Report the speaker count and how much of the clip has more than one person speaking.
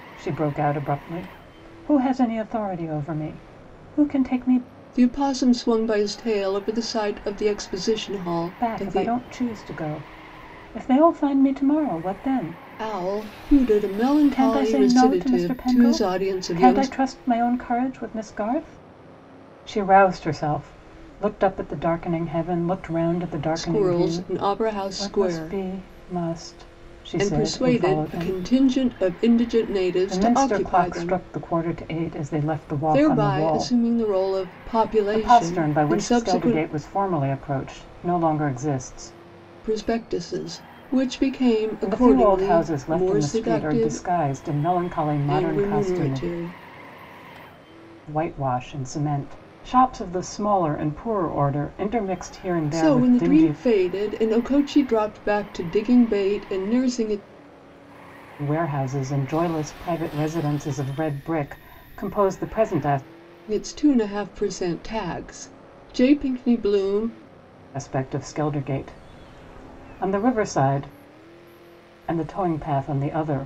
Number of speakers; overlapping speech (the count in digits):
2, about 19%